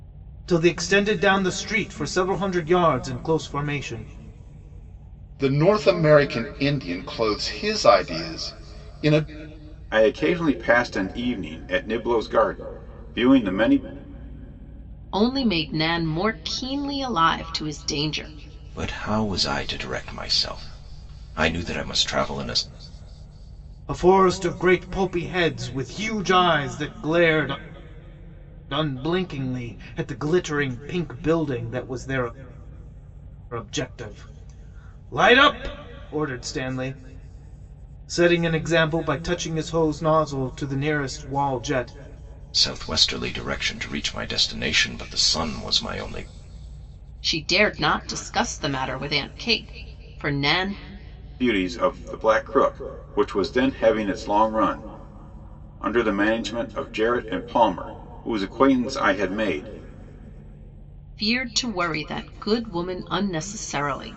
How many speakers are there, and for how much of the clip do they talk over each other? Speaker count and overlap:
five, no overlap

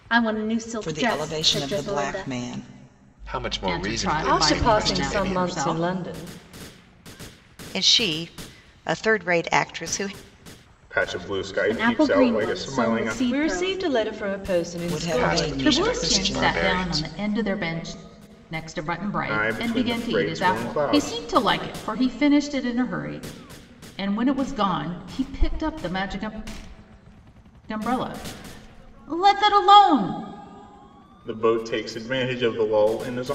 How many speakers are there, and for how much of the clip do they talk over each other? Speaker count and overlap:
seven, about 30%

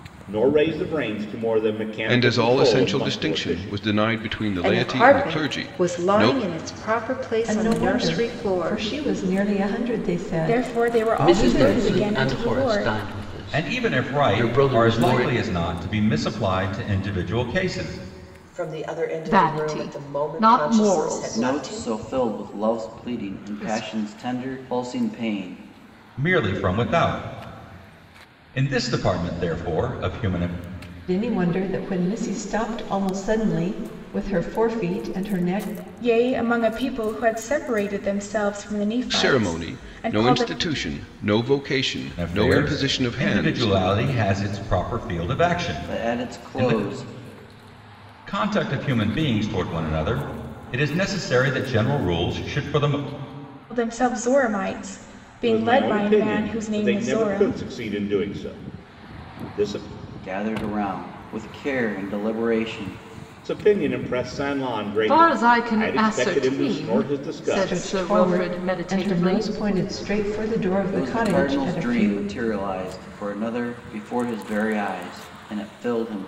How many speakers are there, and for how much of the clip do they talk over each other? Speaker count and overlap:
ten, about 34%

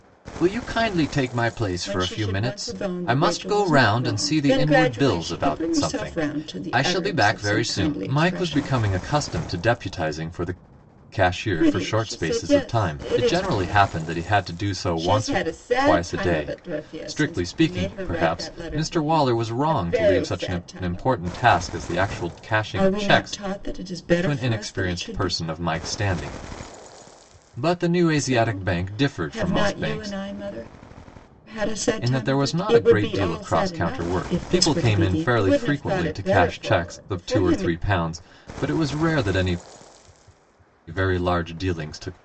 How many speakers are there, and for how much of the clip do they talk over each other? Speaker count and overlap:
two, about 58%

